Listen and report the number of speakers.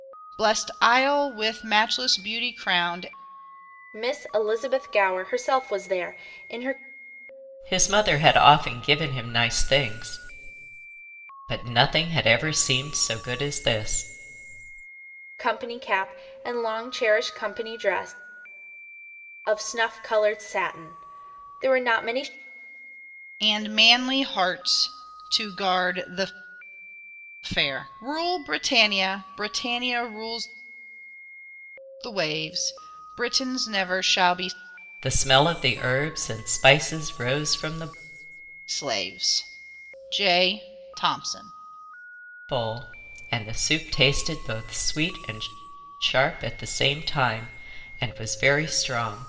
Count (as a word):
three